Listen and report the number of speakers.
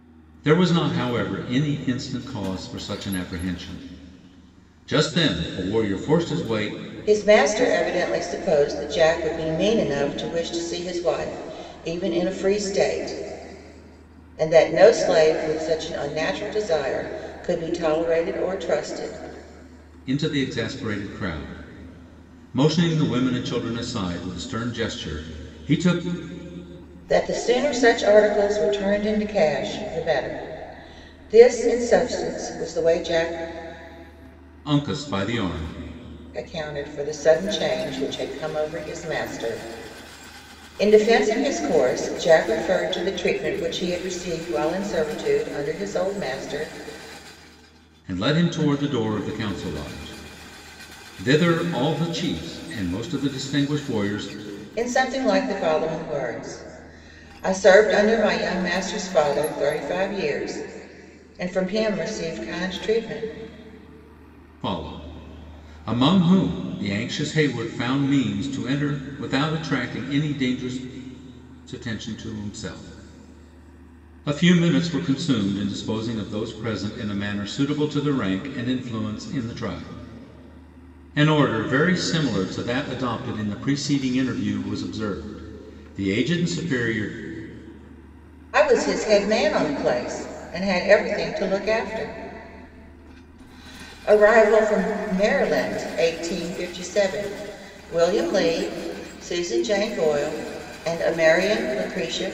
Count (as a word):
two